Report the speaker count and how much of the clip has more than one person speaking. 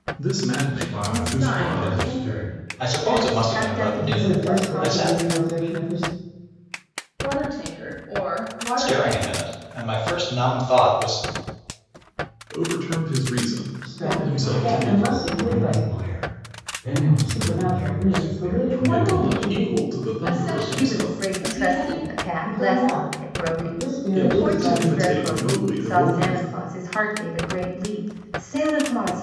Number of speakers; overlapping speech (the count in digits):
6, about 53%